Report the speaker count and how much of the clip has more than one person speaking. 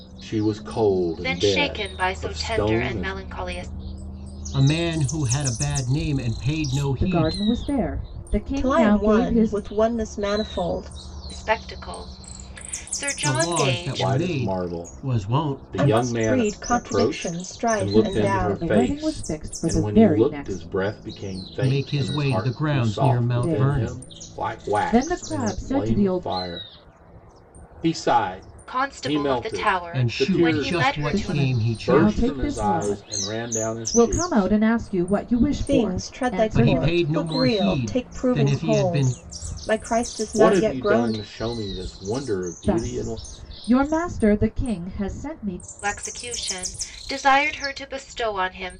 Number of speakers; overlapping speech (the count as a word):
five, about 53%